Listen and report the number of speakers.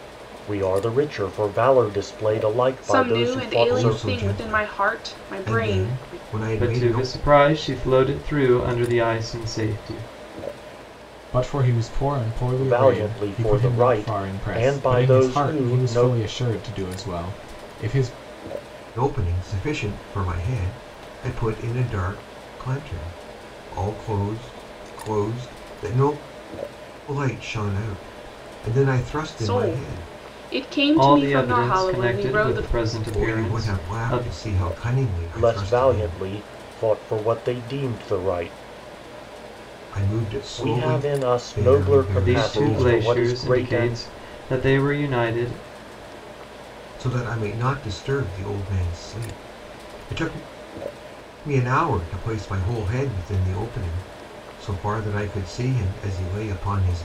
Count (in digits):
5